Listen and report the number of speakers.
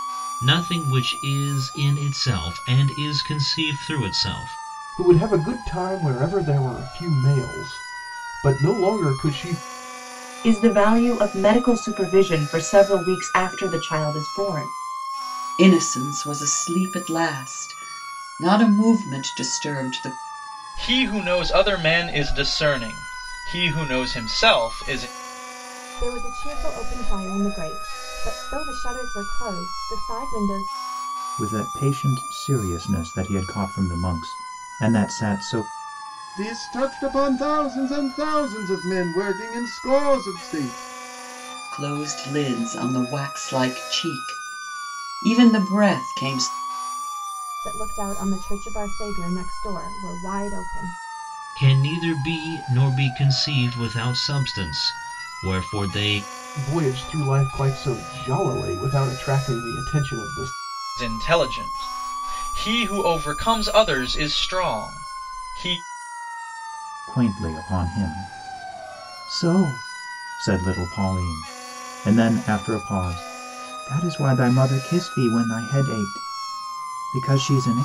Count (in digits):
8